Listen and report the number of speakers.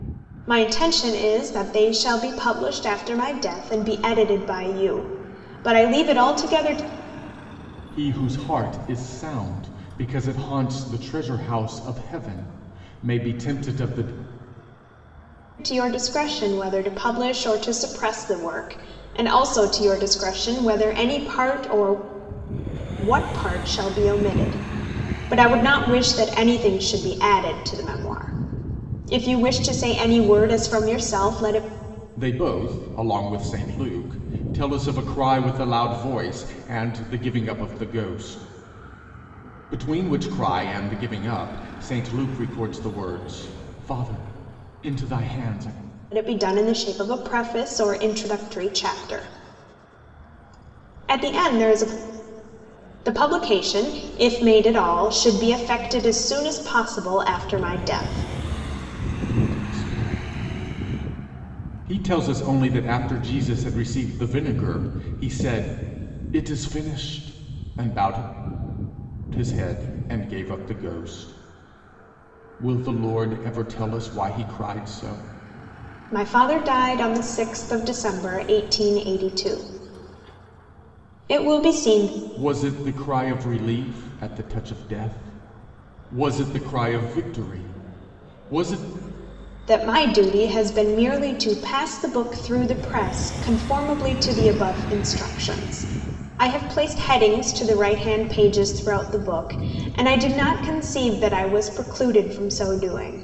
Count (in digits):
2